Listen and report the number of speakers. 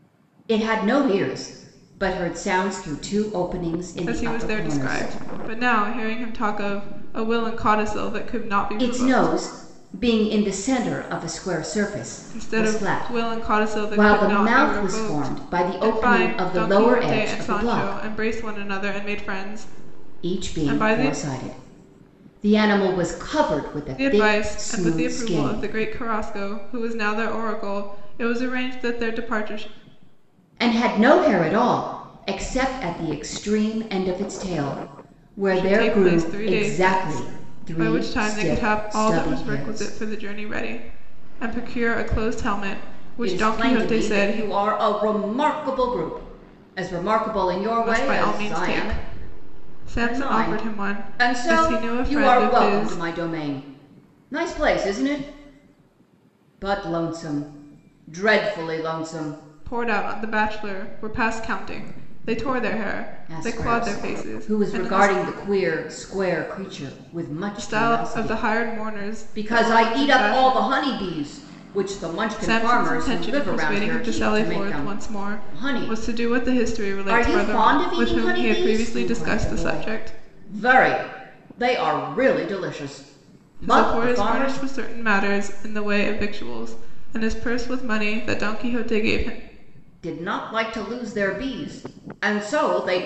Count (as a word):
two